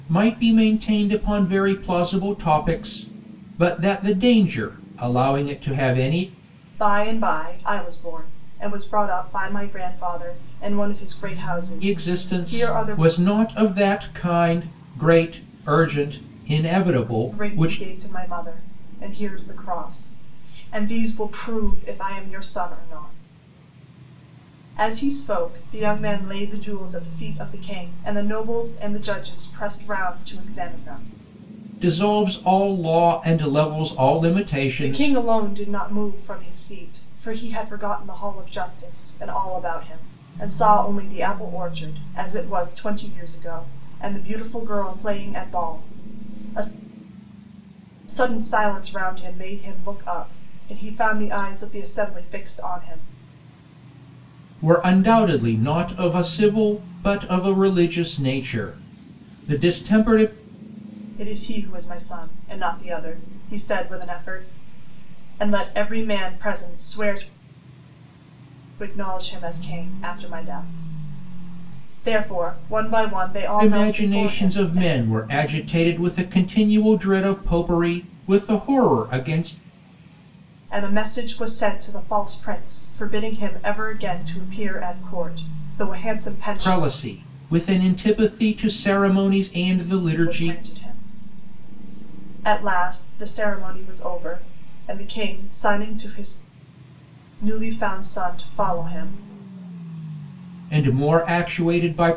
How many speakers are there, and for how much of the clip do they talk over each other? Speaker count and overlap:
2, about 4%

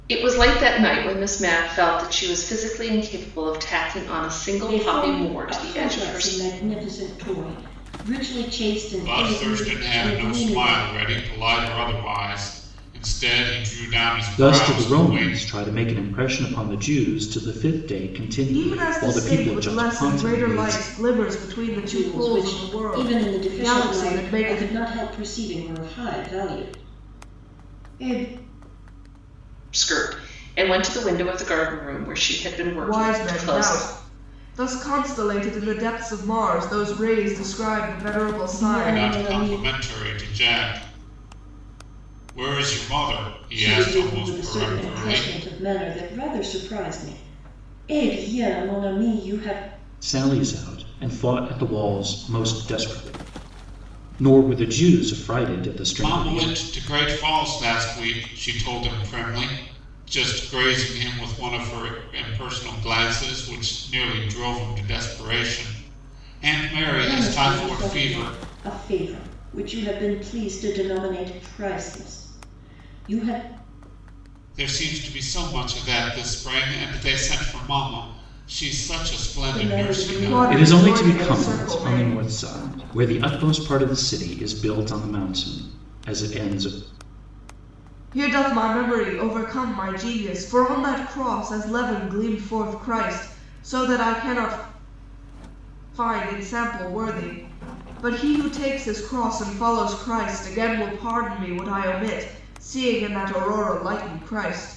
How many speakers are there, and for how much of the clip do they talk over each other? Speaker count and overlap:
5, about 18%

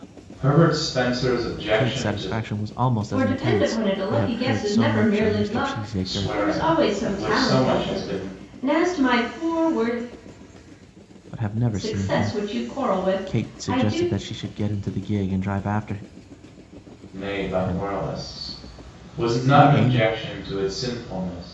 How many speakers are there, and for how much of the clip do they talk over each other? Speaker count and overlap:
3, about 49%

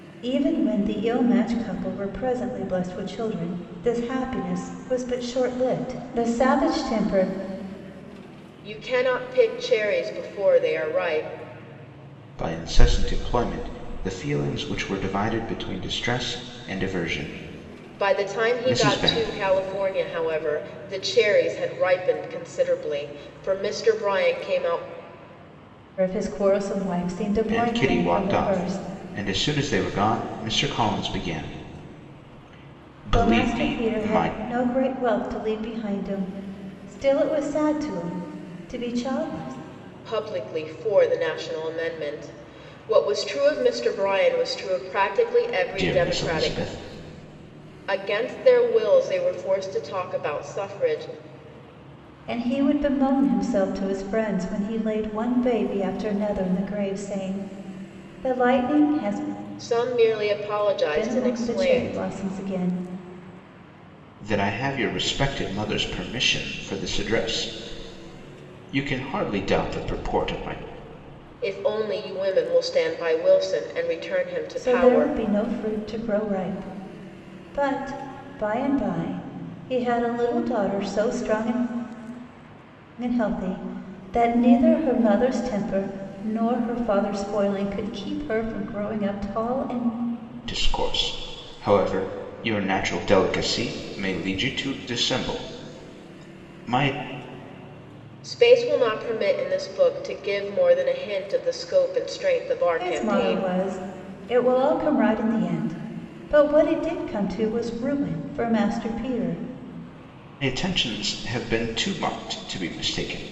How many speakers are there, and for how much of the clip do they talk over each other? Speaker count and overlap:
3, about 7%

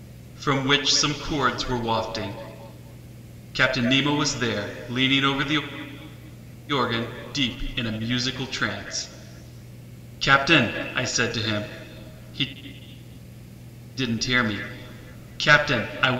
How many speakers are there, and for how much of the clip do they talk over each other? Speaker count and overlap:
1, no overlap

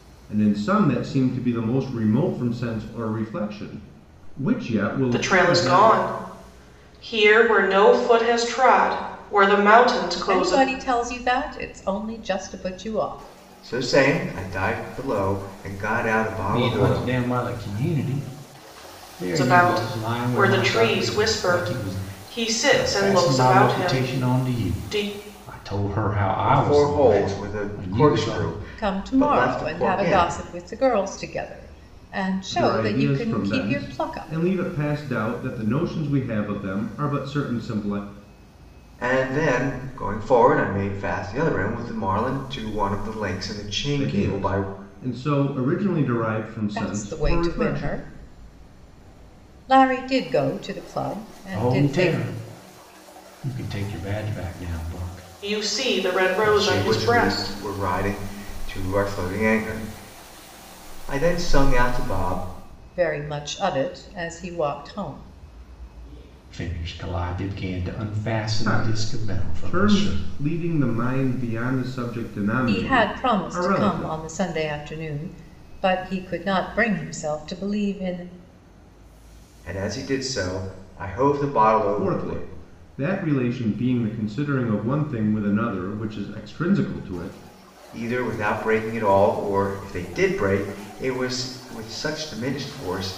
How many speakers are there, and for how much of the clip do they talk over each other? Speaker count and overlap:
5, about 23%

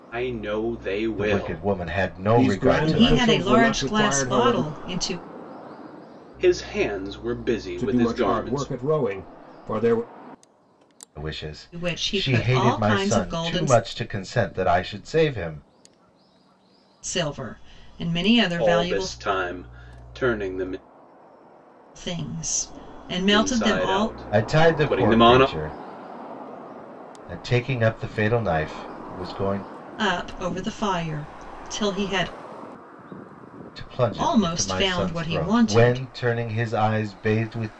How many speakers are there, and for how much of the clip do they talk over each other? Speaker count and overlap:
4, about 28%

